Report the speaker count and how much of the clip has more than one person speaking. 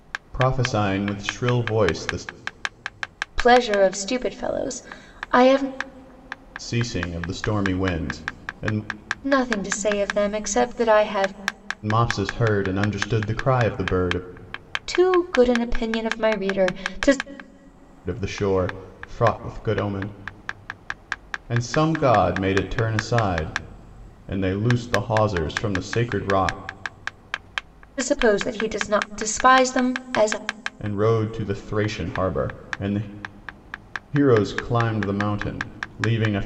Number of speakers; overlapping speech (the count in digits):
2, no overlap